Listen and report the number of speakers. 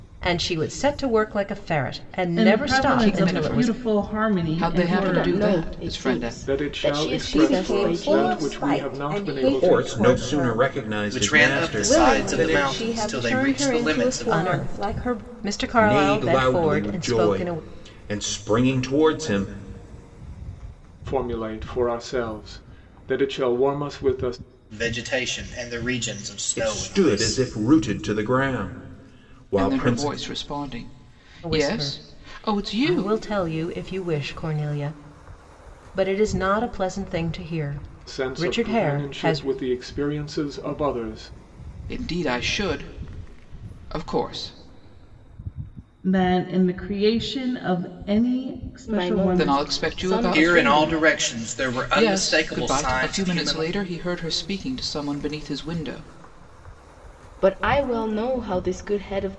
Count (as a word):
eight